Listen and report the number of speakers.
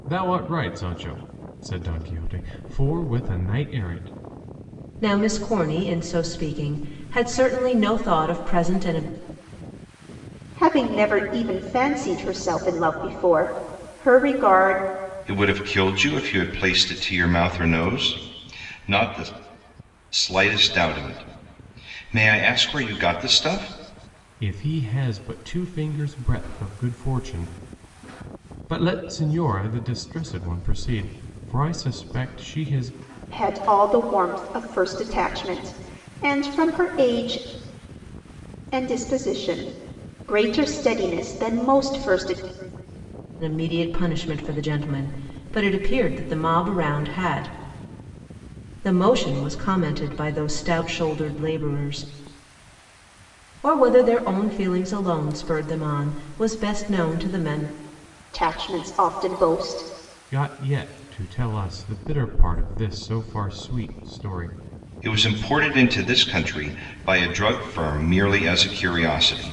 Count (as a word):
four